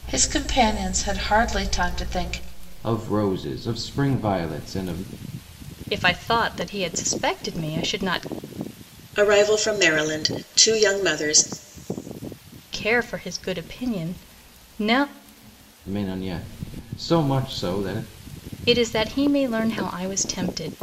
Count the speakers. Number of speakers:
4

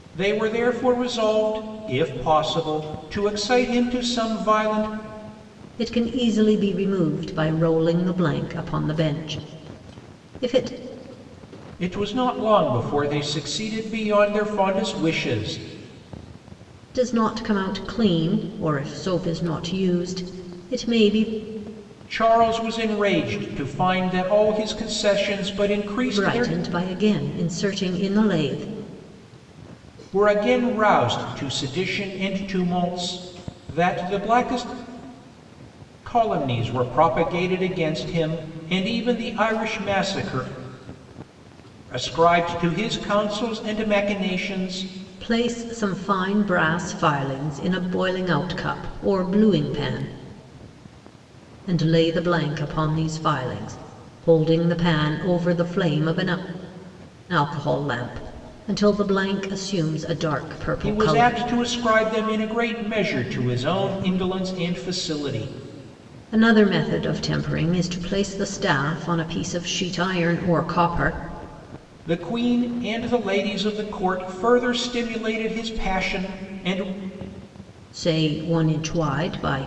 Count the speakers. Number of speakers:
2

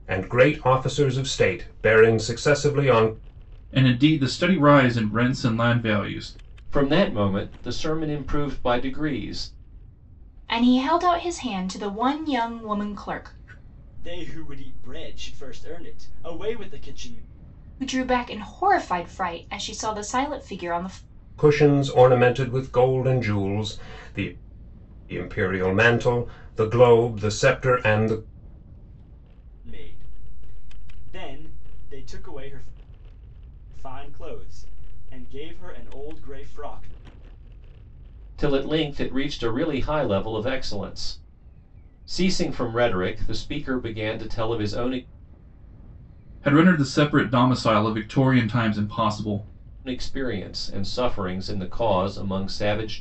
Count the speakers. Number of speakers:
5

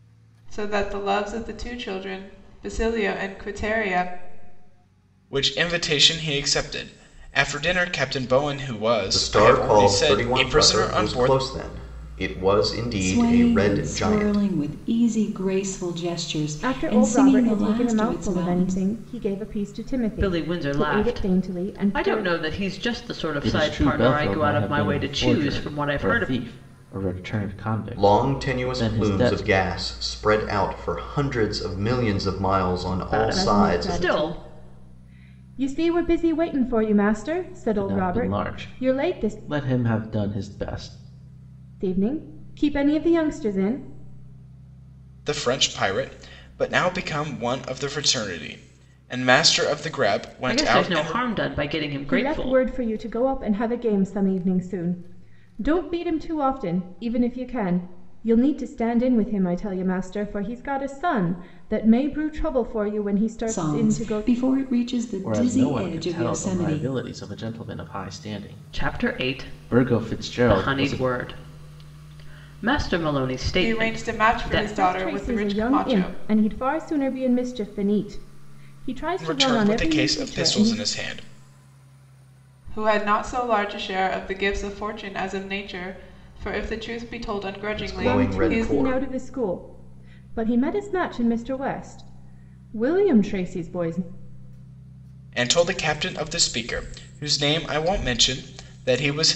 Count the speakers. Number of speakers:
7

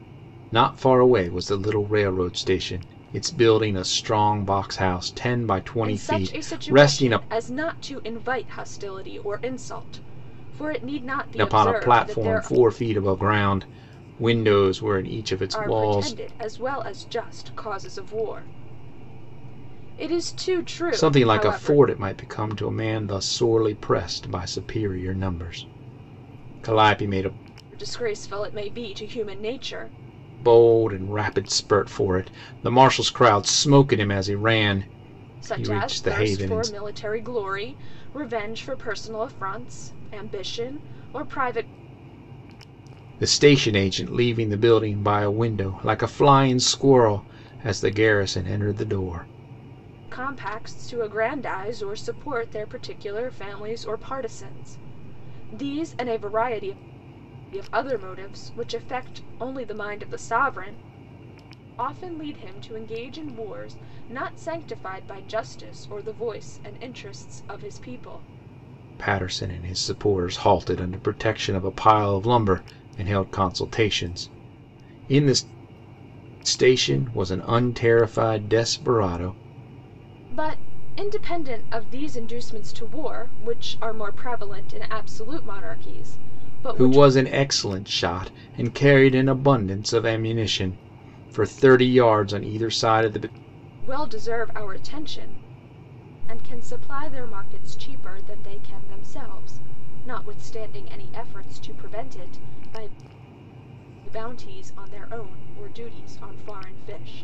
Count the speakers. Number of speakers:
2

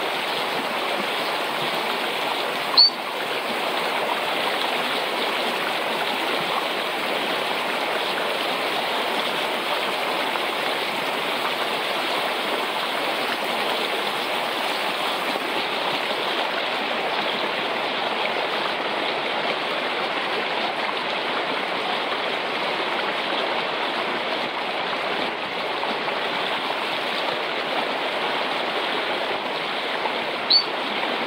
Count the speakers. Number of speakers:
0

